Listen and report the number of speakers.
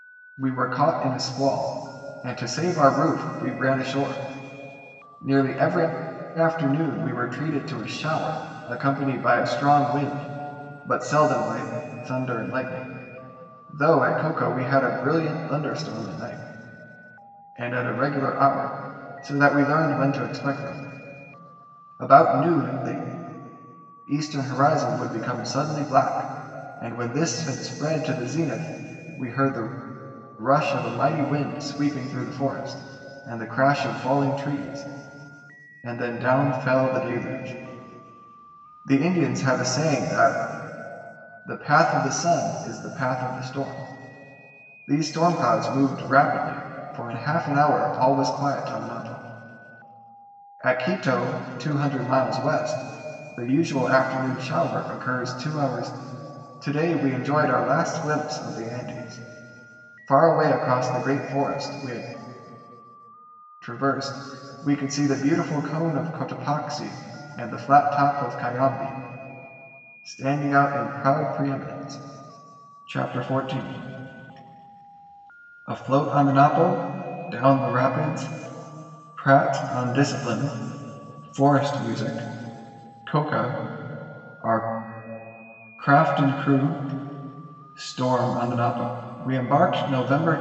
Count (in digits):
1